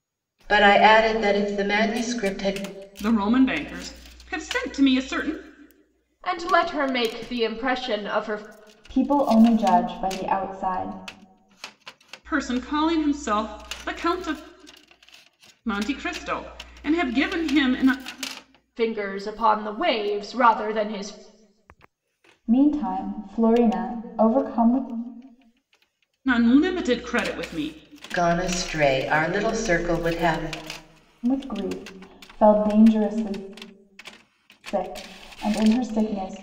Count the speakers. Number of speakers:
4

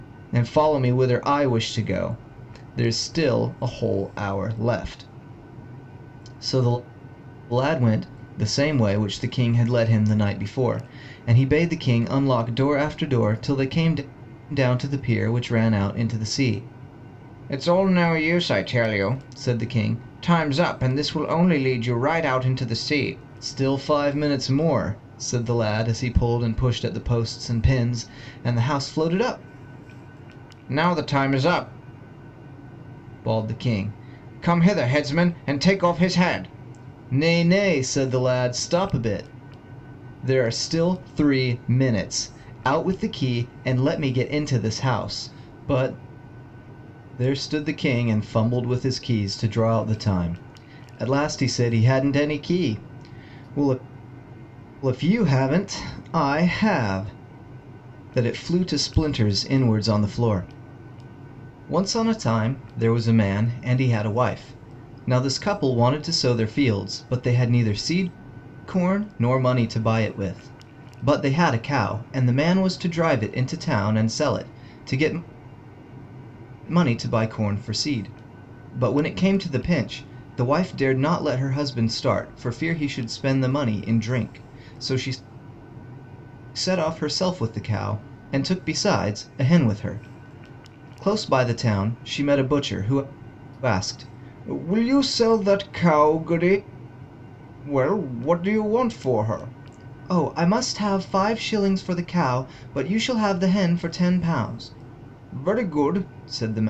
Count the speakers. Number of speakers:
1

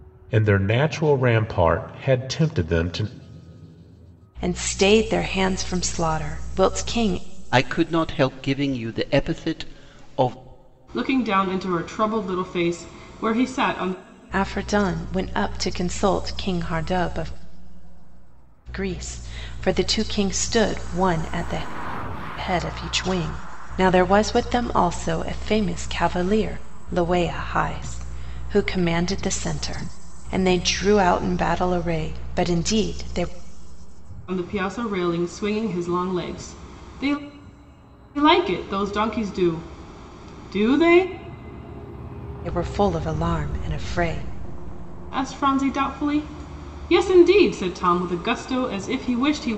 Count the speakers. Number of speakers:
4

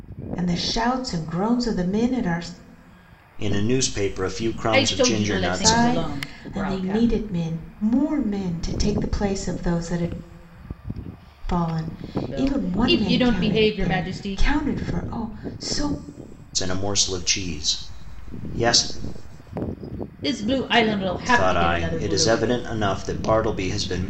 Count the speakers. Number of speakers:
3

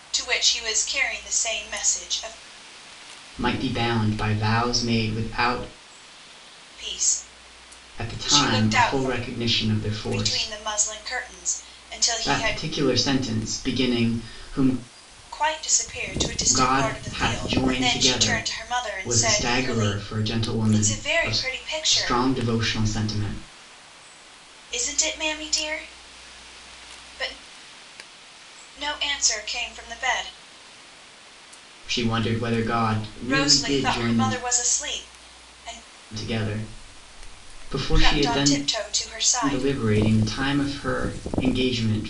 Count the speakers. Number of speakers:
2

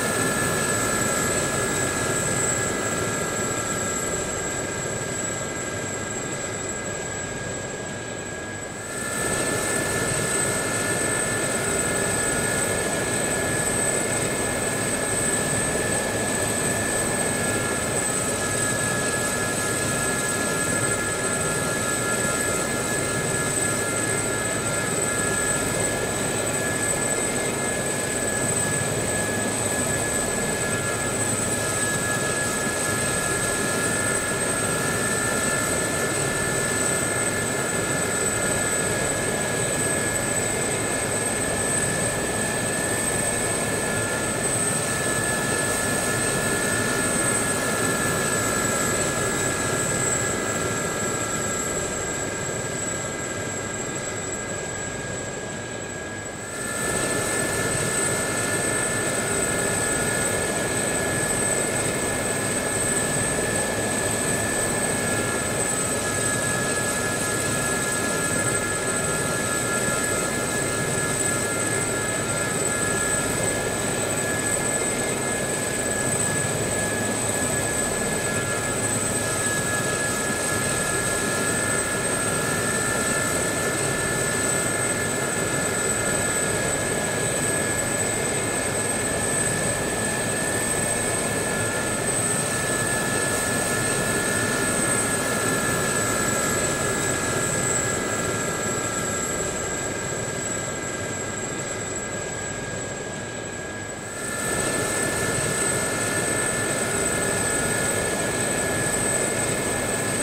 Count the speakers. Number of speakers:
0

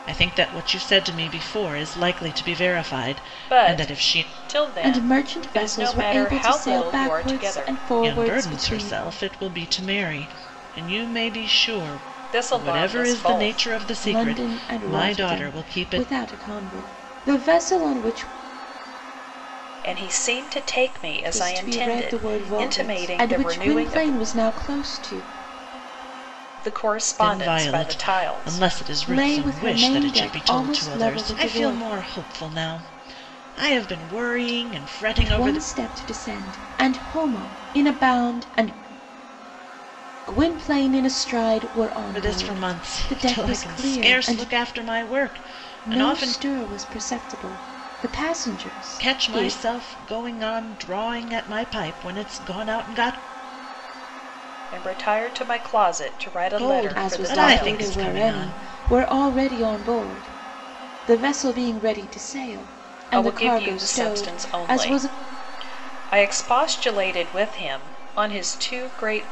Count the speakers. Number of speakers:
3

